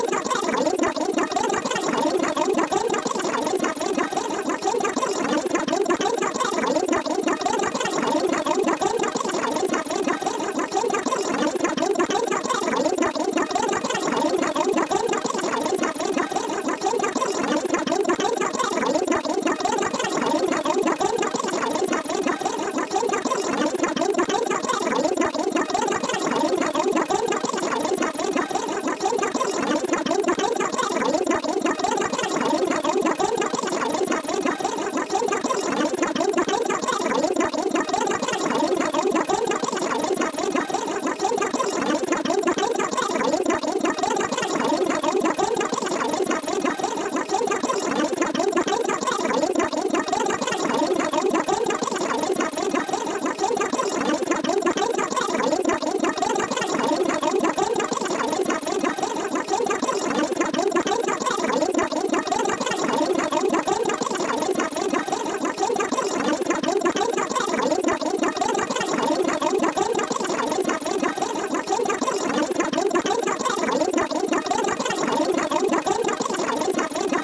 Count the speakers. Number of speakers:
zero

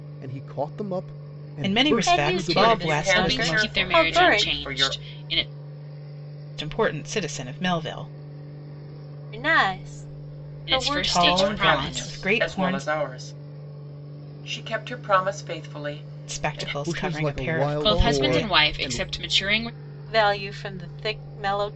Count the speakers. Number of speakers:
five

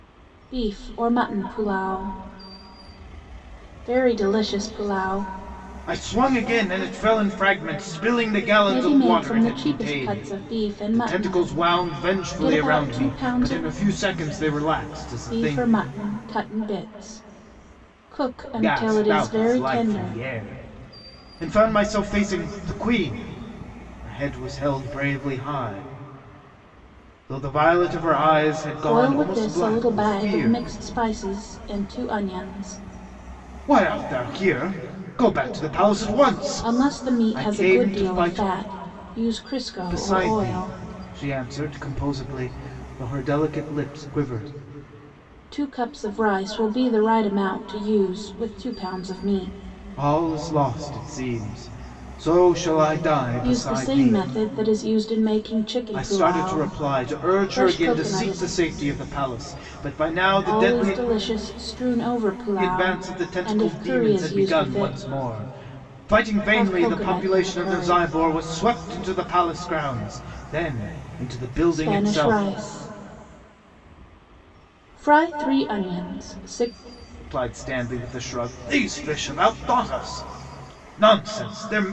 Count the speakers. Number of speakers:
two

